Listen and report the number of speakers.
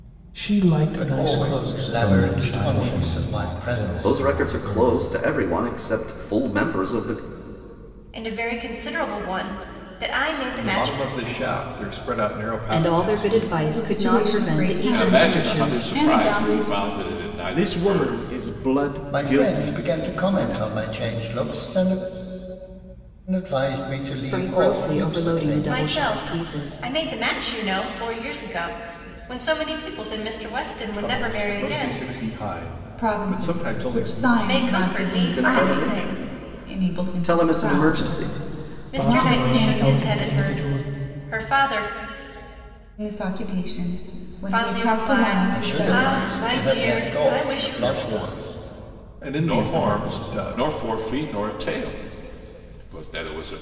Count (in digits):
10